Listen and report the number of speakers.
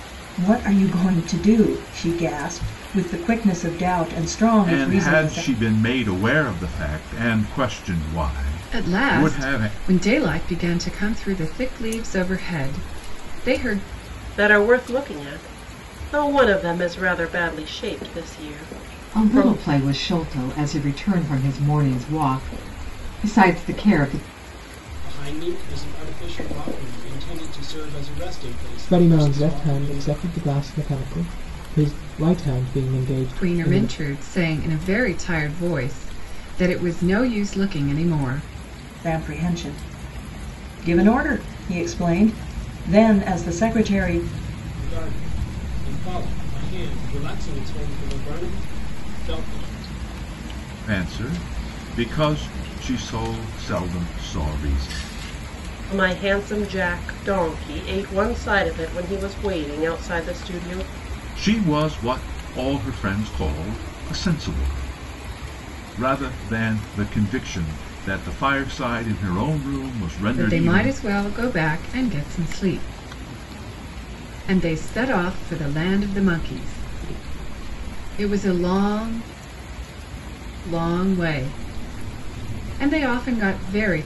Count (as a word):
seven